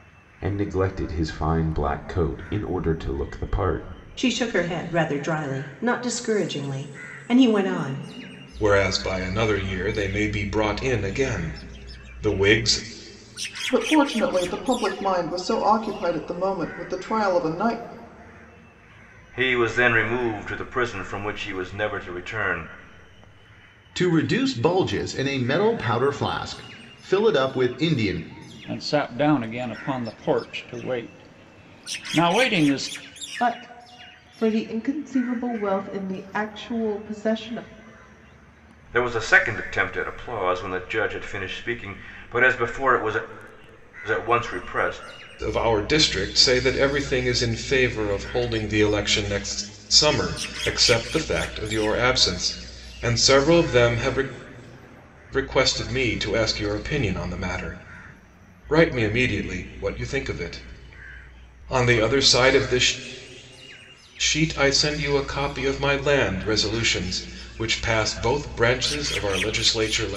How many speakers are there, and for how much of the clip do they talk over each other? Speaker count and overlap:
8, no overlap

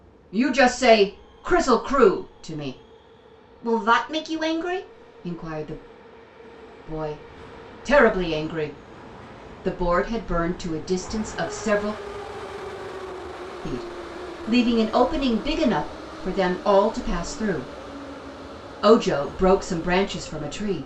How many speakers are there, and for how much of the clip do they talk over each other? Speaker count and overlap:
1, no overlap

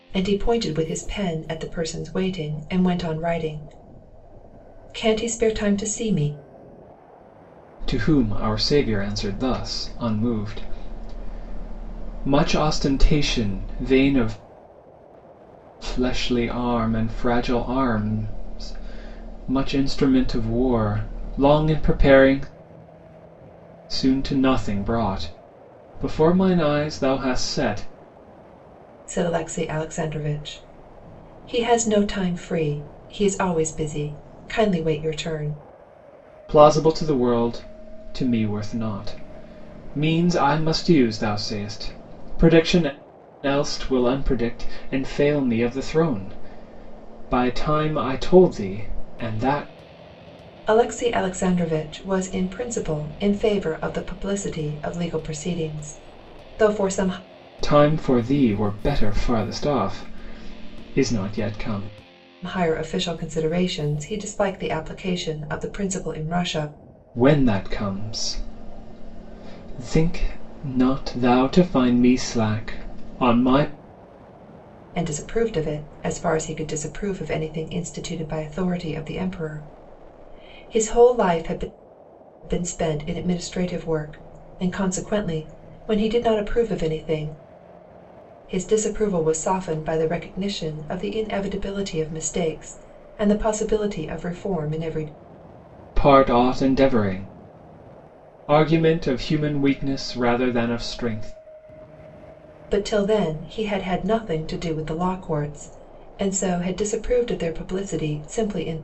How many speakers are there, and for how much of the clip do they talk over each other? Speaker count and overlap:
2, no overlap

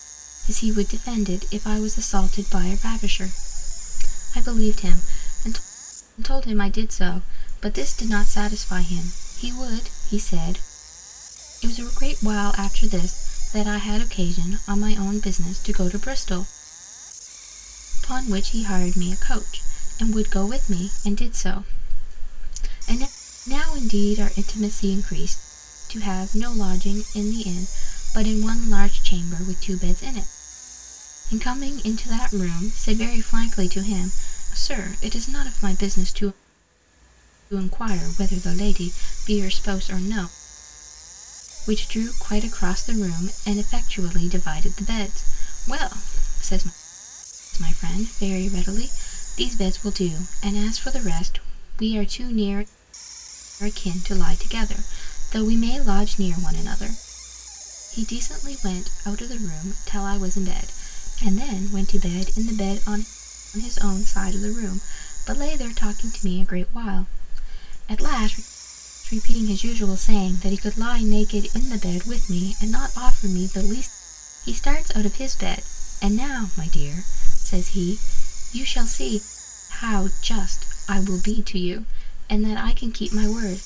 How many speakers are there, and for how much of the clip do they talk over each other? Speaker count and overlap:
1, no overlap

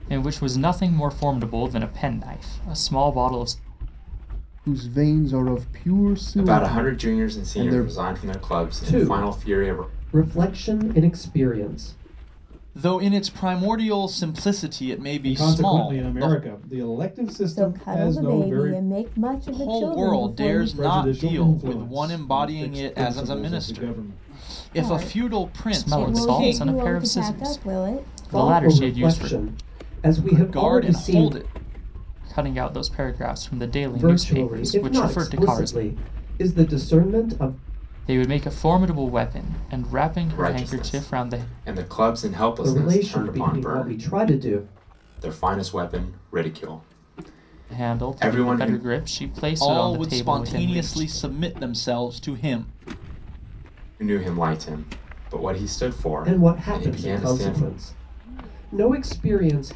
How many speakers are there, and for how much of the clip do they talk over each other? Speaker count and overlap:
7, about 41%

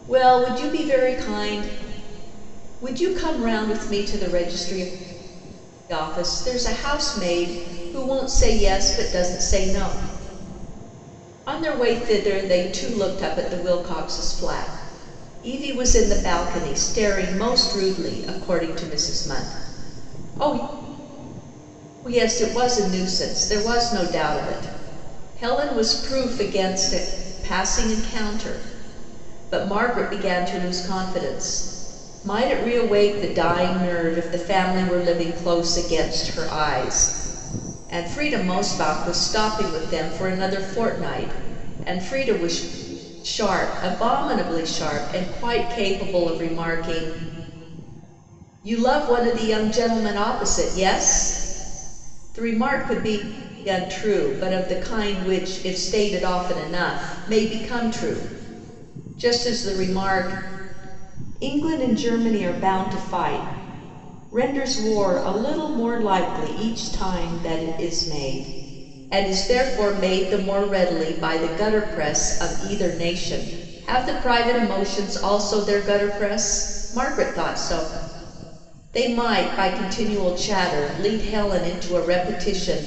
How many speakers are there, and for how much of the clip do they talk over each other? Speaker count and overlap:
1, no overlap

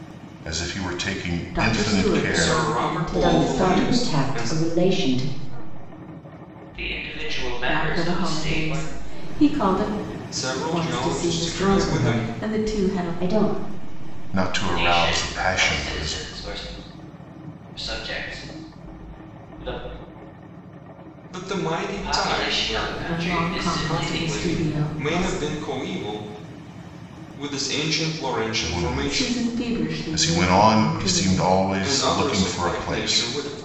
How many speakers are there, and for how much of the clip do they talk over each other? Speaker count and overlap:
6, about 56%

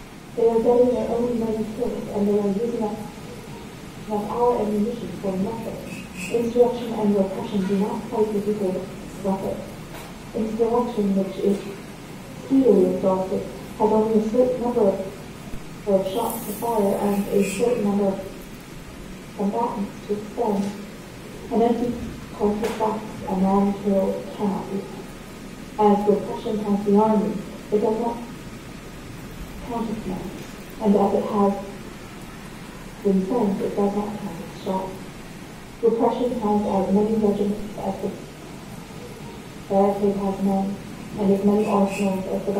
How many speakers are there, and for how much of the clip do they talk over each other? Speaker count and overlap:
1, no overlap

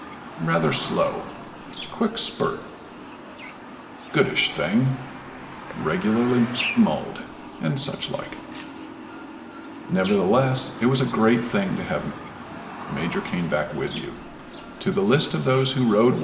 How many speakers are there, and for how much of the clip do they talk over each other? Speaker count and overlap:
1, no overlap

